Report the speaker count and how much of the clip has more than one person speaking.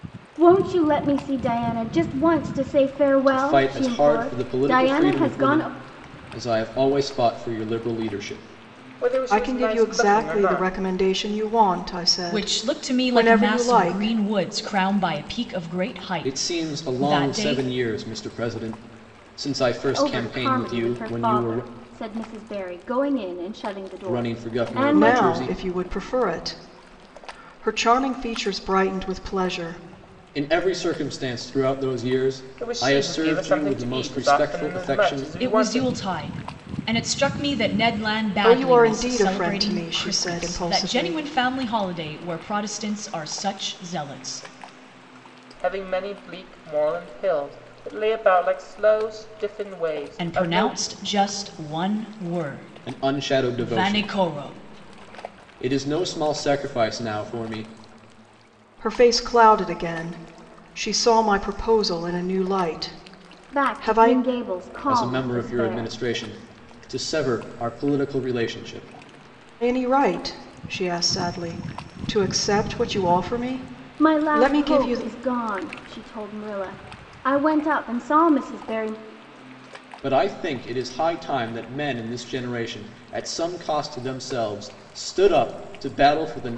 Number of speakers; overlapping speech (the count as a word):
five, about 25%